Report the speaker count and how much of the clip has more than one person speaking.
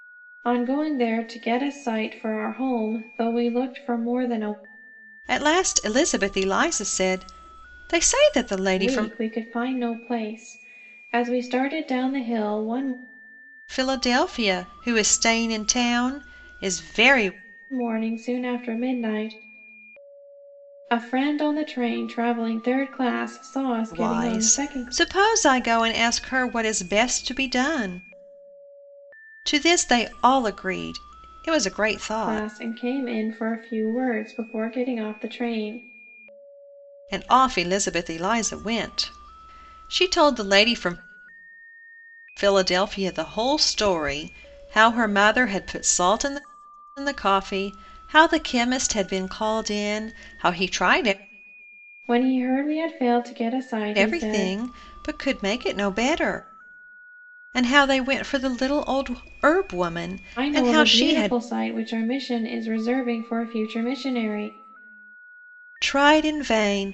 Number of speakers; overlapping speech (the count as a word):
two, about 5%